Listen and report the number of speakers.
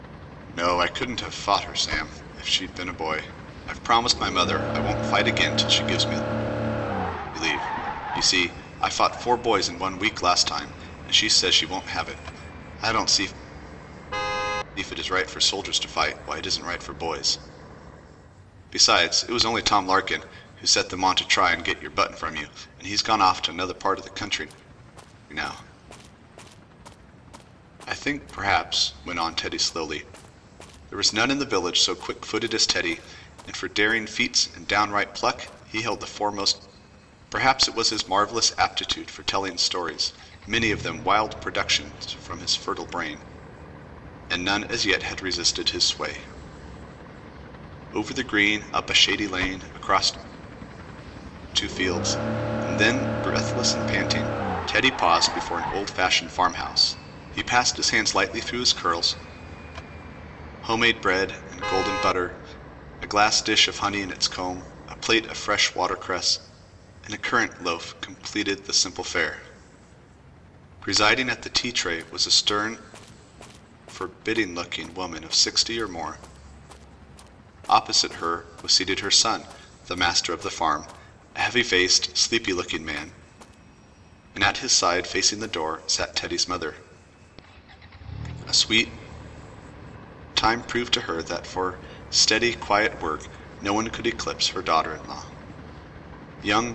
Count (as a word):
one